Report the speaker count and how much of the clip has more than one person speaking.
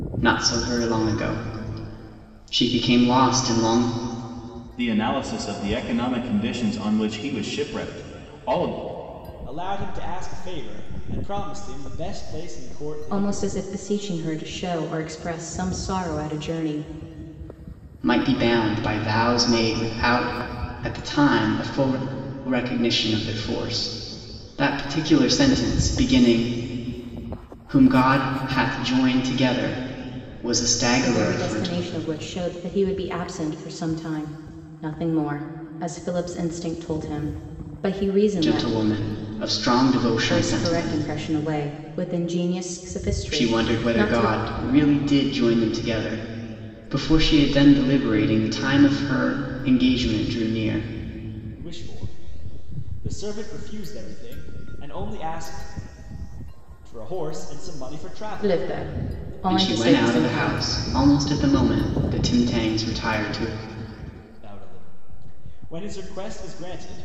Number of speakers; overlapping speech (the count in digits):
4, about 7%